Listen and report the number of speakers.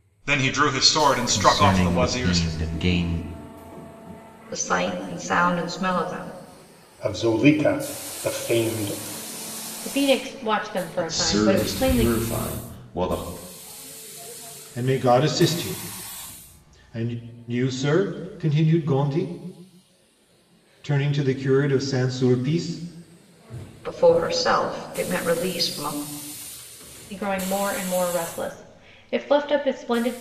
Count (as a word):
seven